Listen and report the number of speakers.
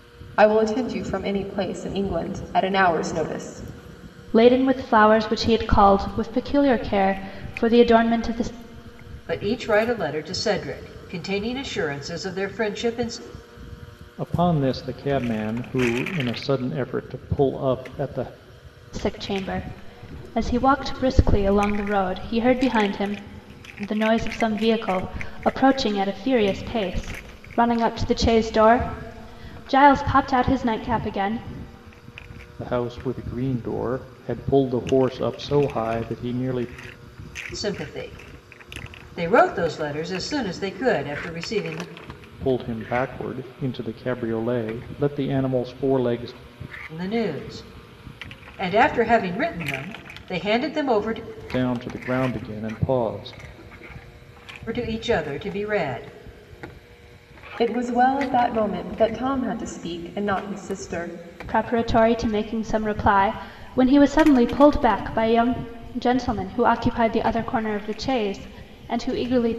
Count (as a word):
four